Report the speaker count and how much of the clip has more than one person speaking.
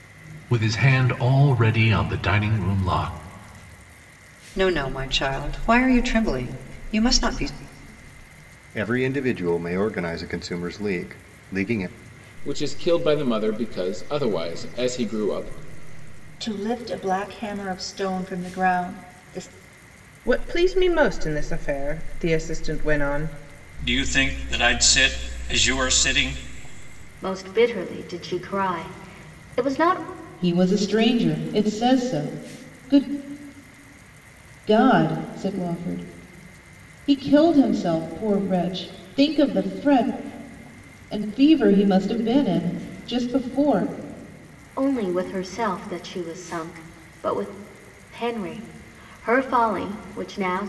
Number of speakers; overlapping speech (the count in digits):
9, no overlap